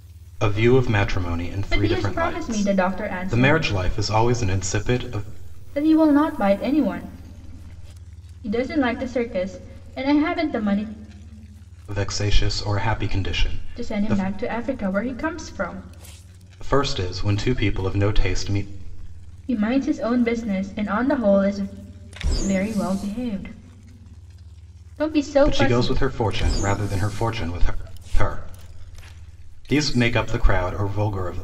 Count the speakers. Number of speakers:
2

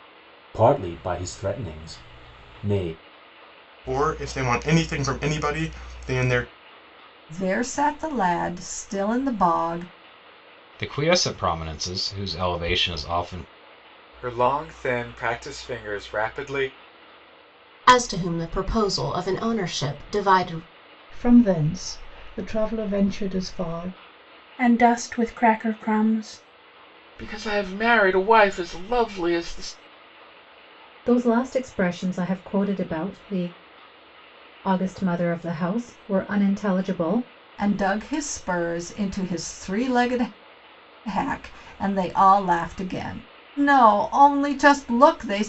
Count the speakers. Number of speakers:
10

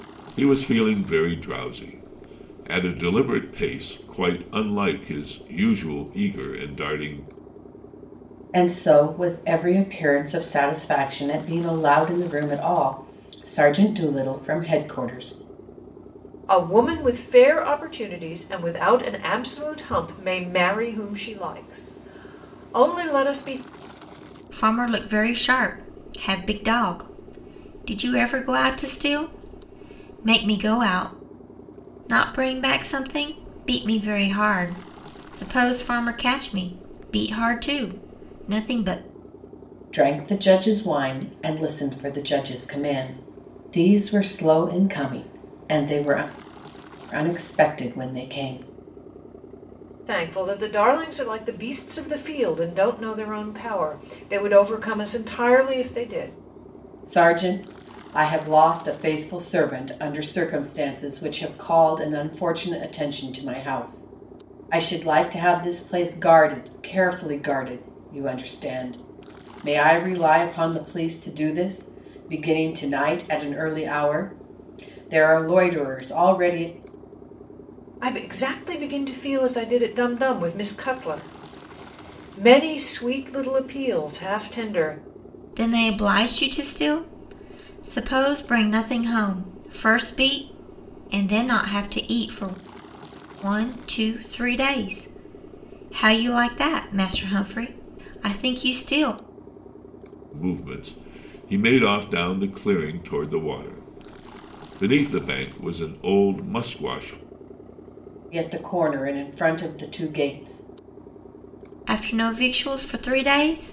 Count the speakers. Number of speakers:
4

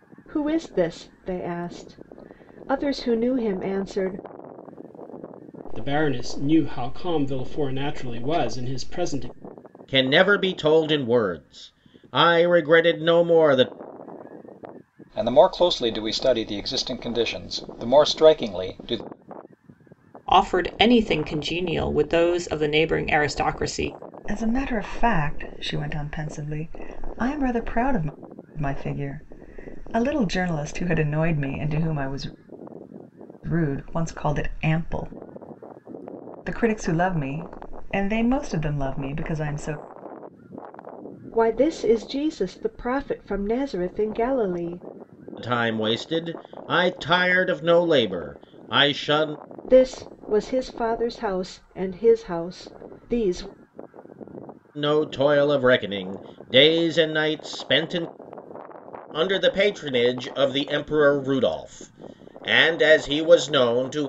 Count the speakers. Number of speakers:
6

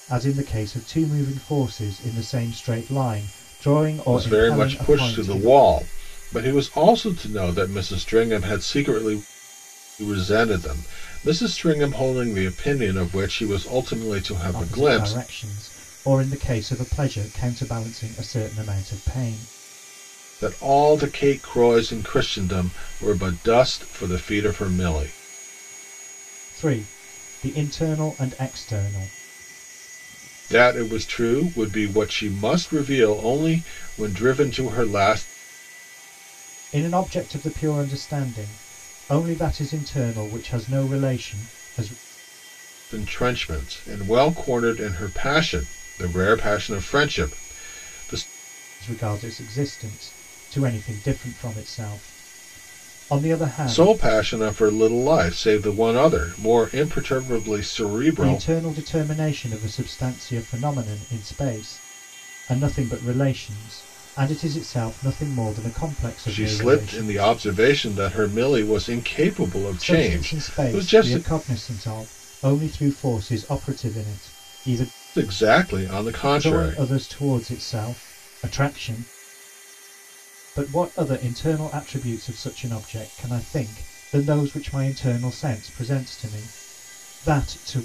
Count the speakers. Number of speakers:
2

